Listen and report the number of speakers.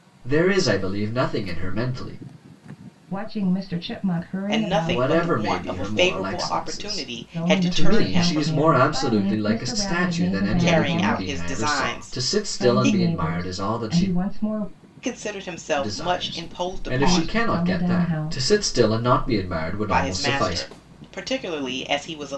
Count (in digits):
3